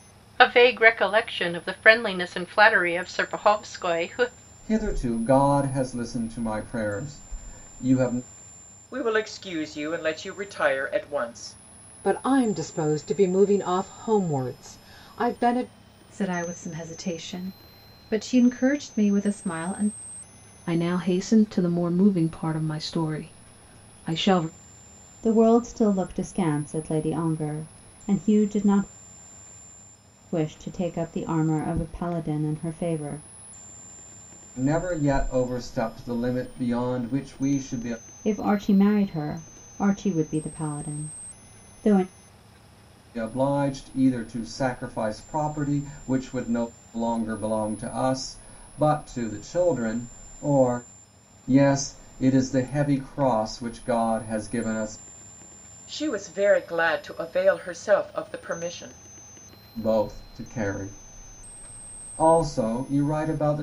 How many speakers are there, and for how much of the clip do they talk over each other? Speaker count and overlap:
7, no overlap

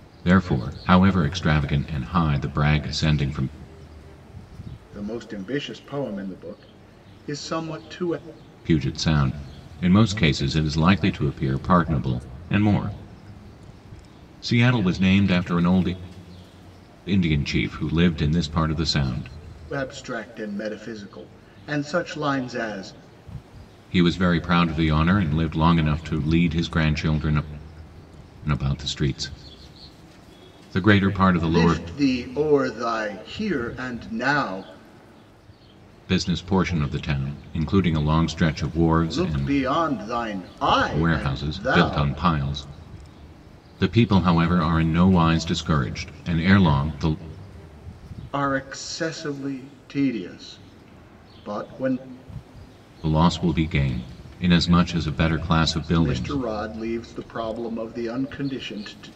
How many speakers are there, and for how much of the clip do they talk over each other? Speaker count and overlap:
2, about 4%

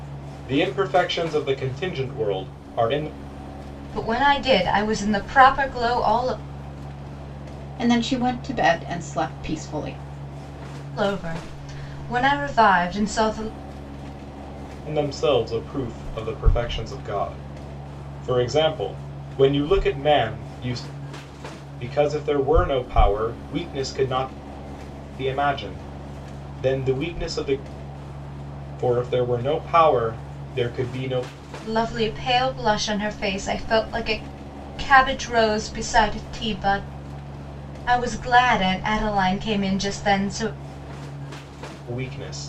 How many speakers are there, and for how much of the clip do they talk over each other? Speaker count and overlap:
3, no overlap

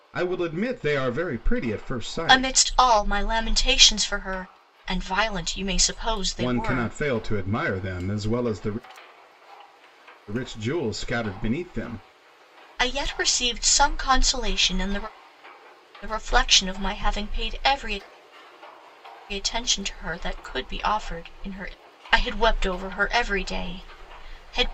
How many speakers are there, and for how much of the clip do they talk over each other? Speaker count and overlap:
2, about 3%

